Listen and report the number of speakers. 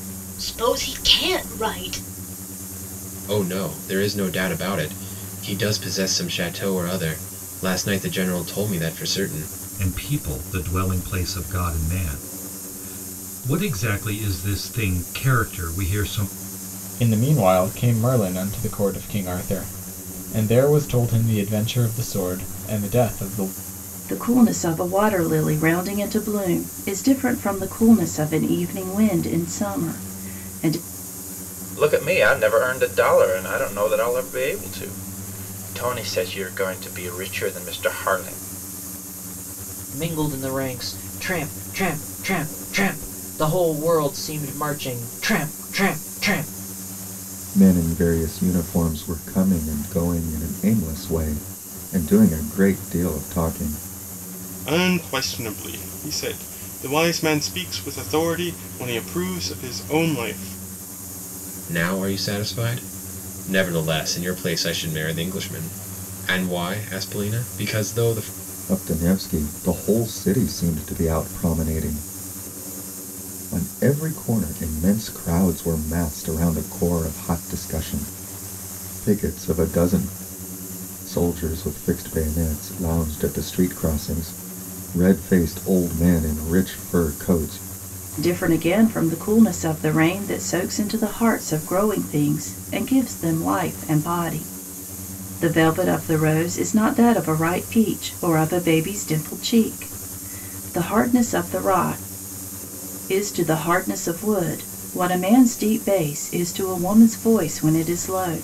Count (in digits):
9